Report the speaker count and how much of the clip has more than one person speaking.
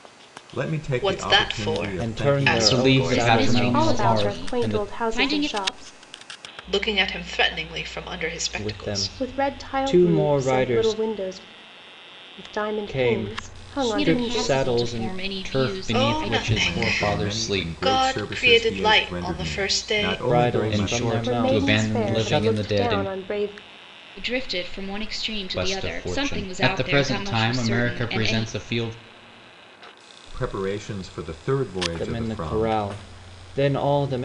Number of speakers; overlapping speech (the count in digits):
6, about 61%